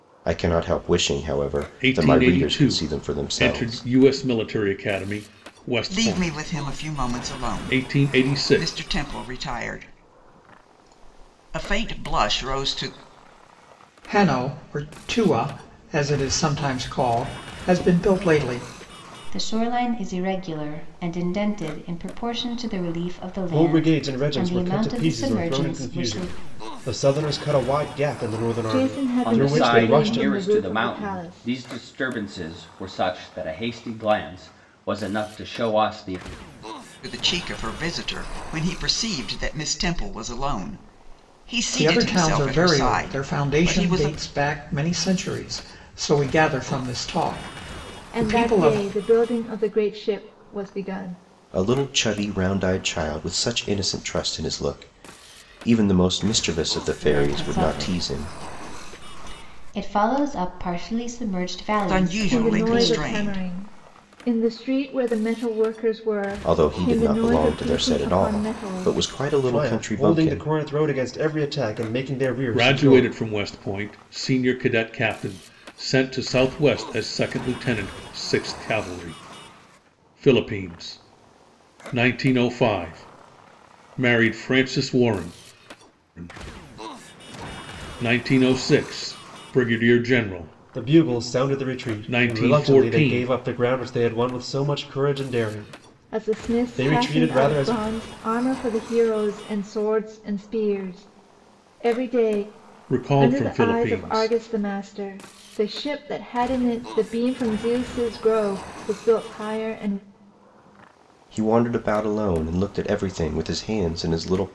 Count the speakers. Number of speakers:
8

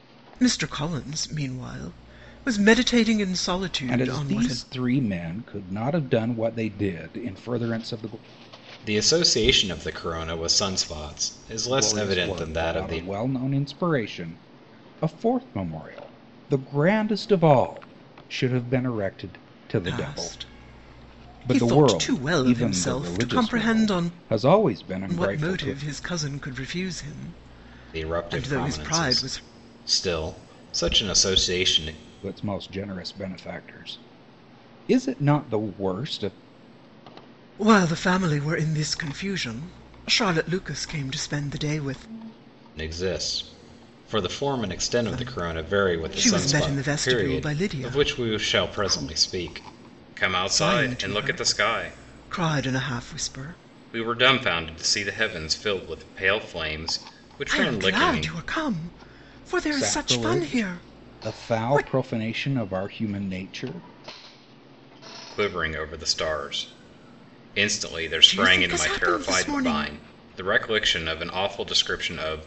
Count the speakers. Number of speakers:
3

